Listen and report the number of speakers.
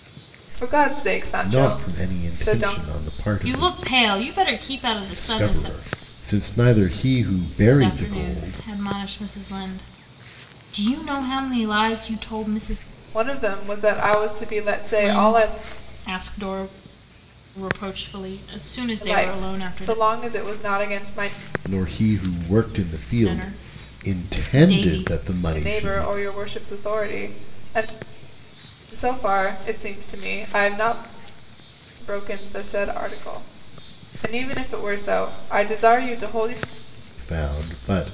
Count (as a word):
three